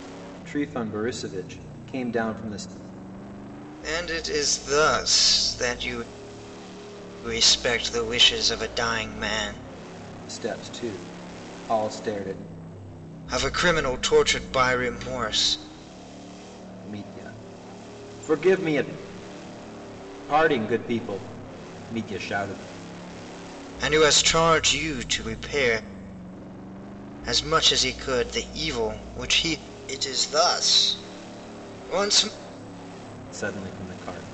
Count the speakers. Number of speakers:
two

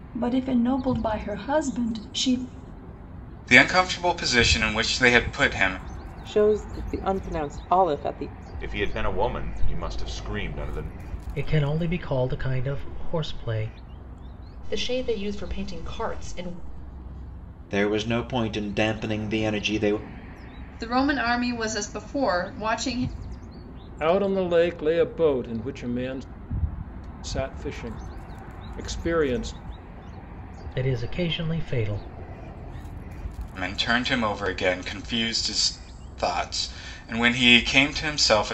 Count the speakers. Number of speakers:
nine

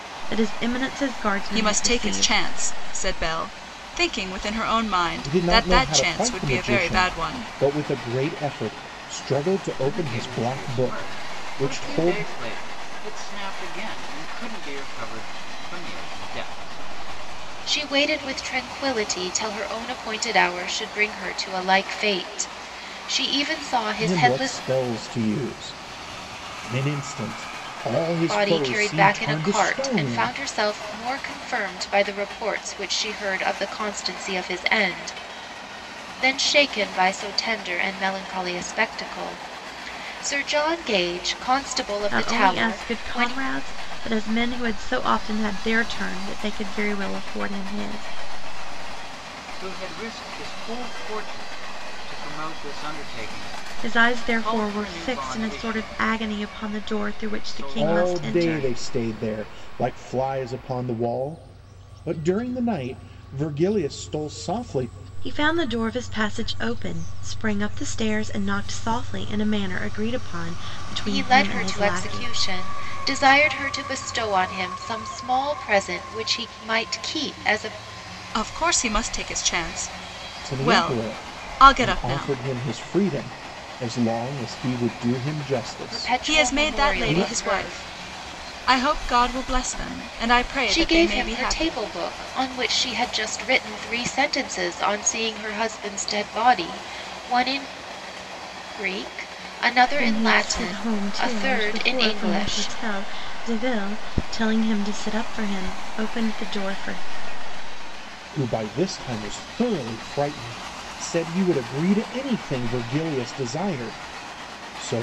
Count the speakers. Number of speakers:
five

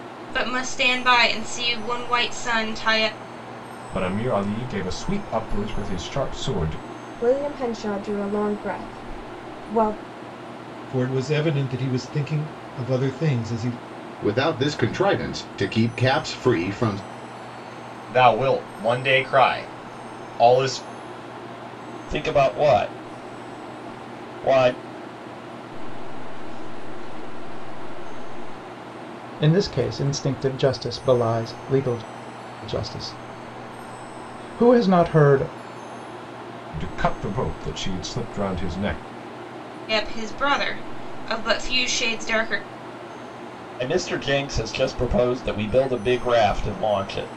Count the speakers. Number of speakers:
nine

